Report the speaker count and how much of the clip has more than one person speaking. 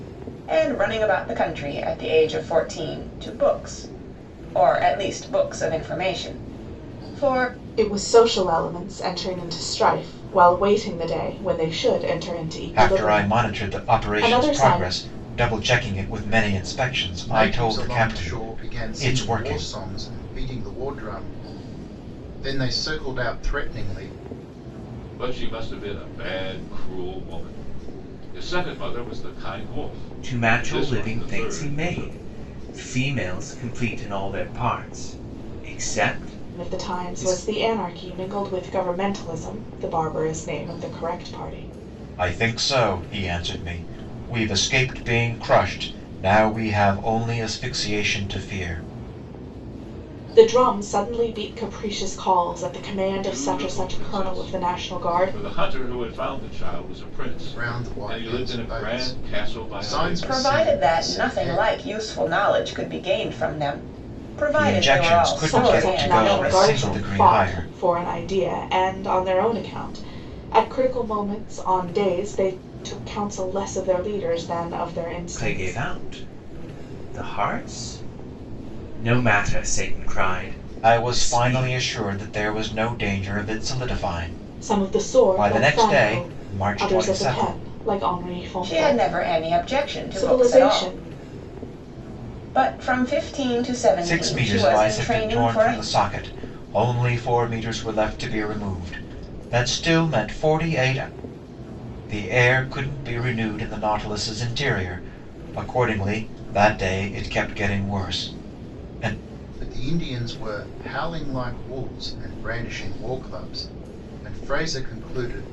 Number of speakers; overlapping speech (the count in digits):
6, about 22%